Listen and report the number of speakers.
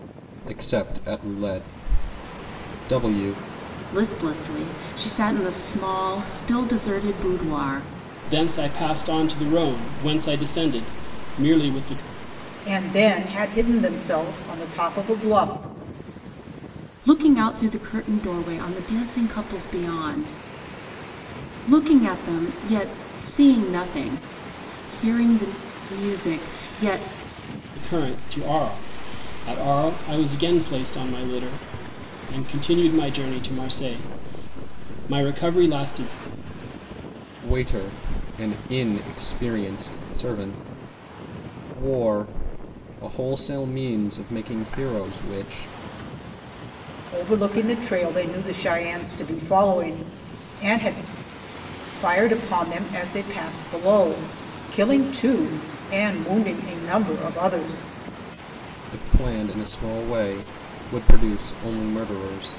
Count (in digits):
4